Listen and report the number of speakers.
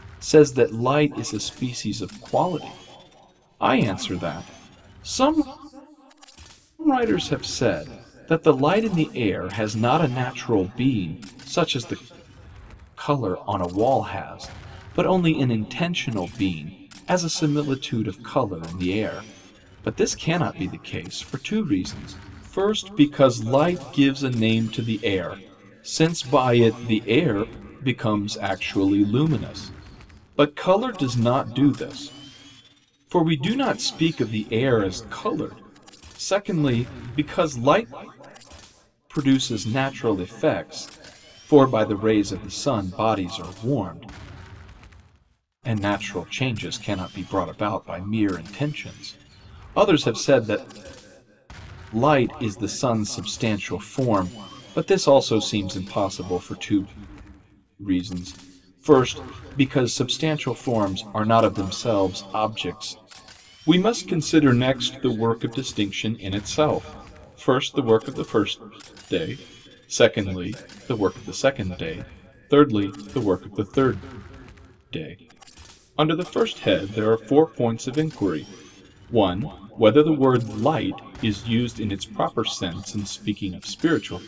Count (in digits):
1